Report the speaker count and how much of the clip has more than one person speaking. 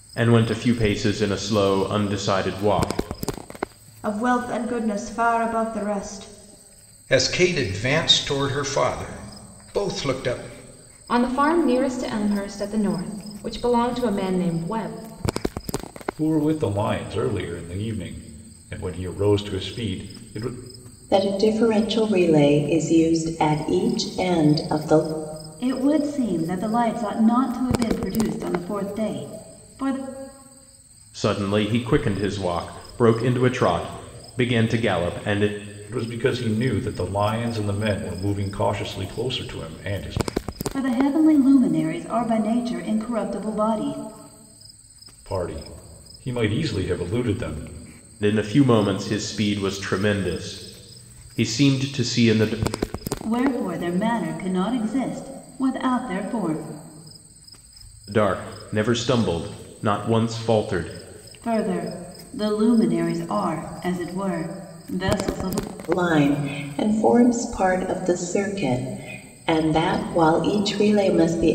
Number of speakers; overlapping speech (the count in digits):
7, no overlap